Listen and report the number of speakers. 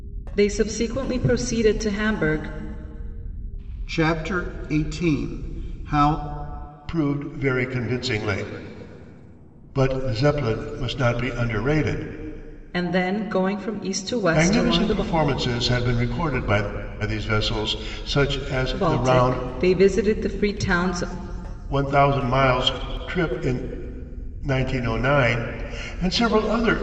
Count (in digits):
3